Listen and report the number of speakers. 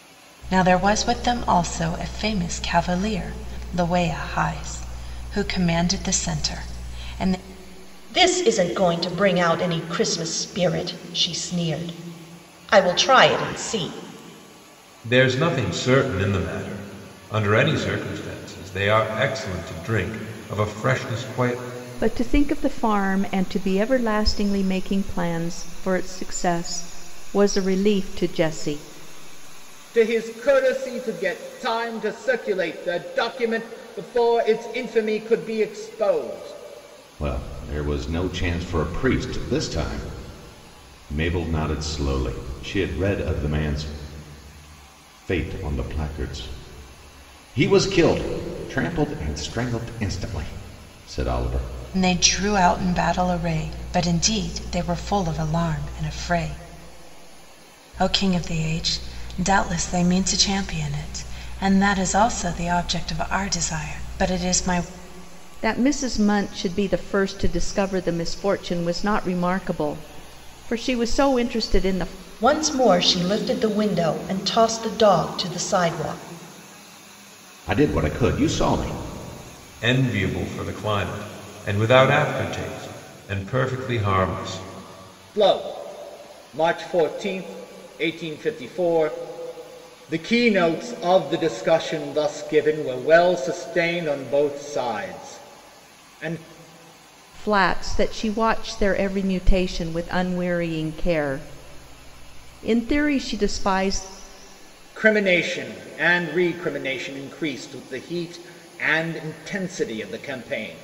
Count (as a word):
six